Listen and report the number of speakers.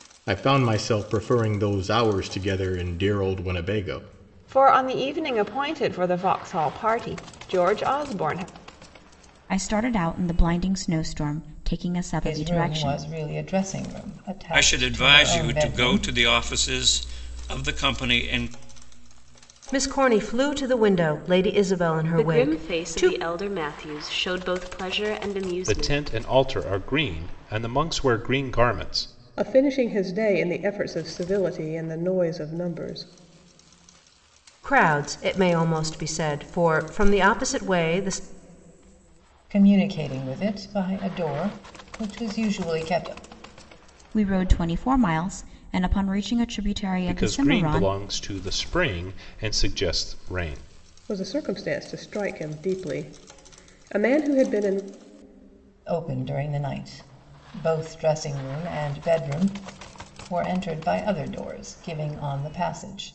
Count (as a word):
nine